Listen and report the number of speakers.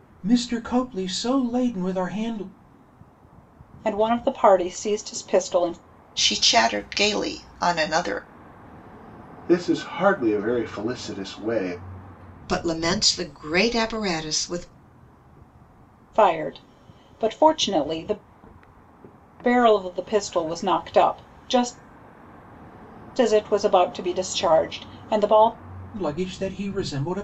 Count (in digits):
5